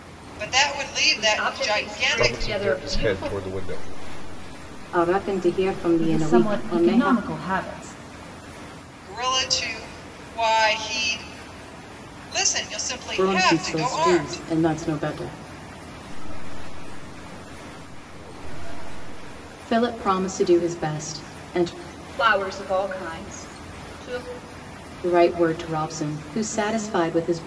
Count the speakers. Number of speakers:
6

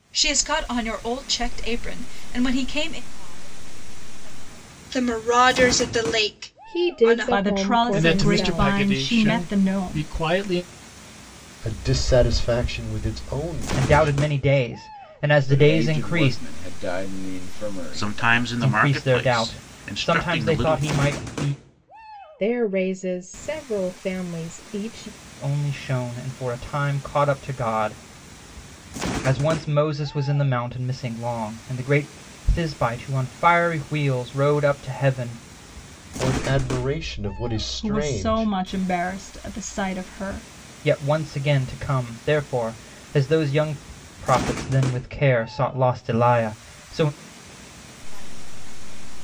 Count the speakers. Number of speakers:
10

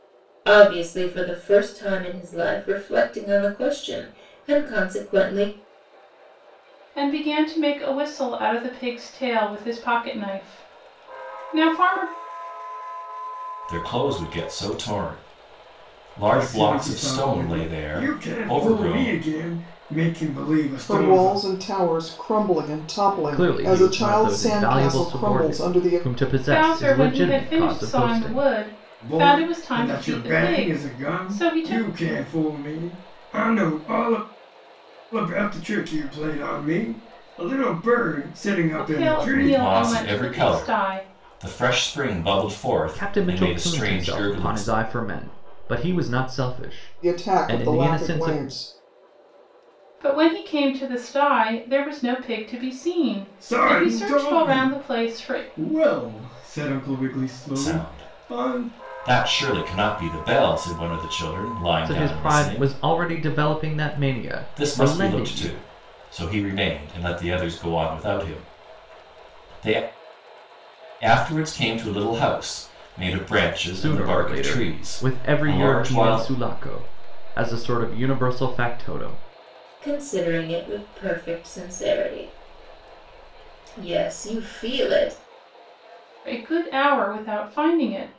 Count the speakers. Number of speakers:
6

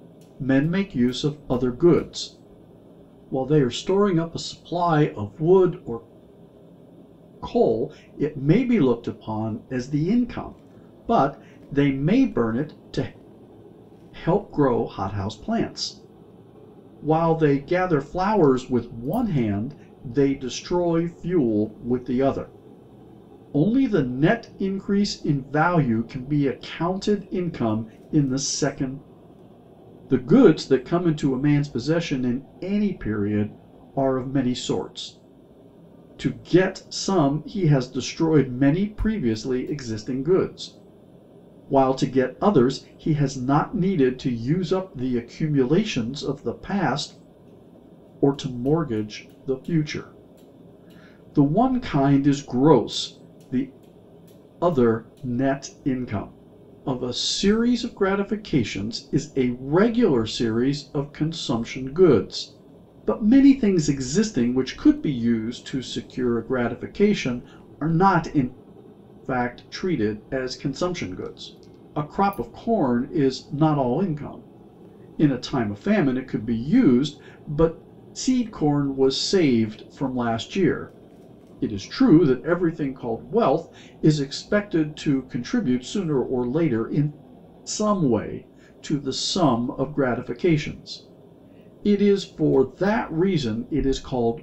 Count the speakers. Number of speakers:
1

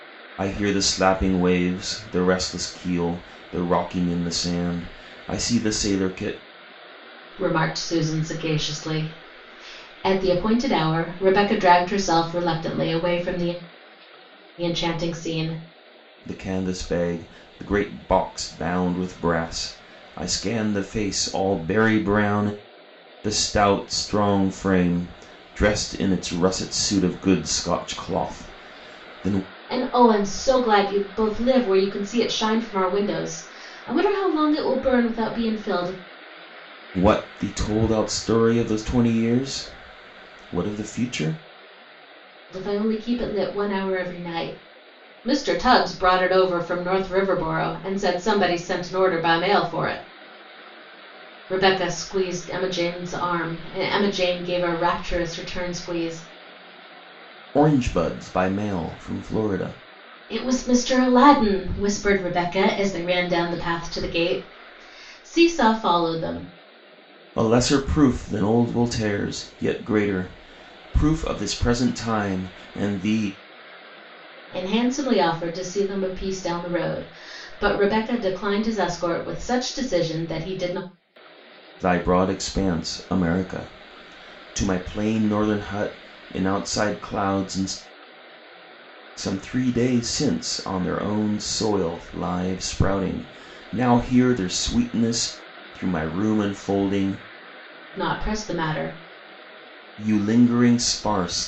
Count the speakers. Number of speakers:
2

